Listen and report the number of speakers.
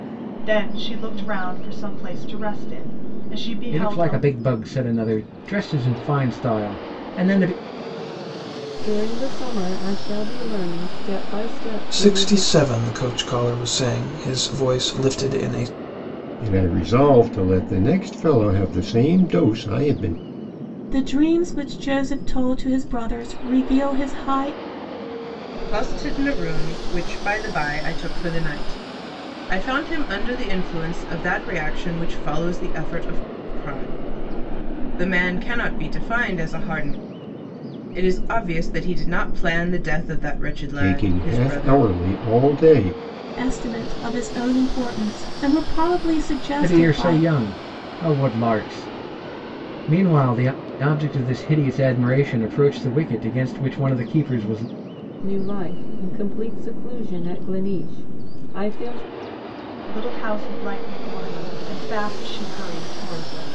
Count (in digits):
7